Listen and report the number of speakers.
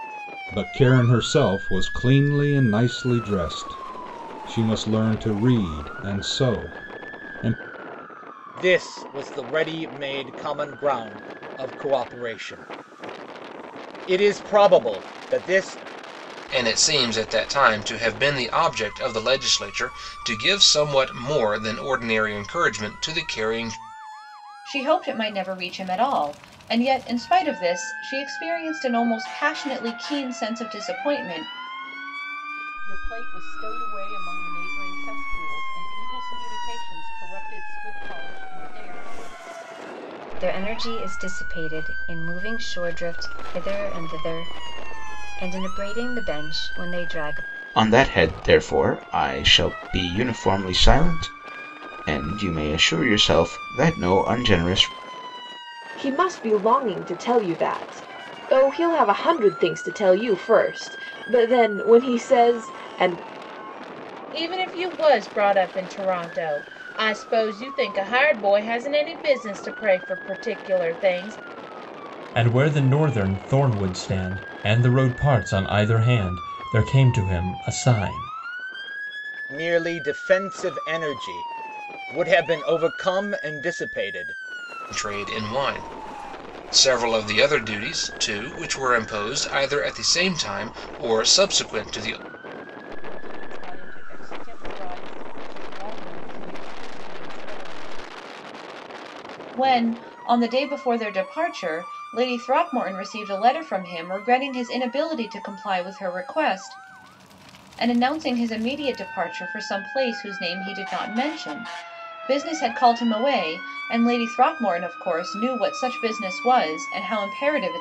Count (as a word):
ten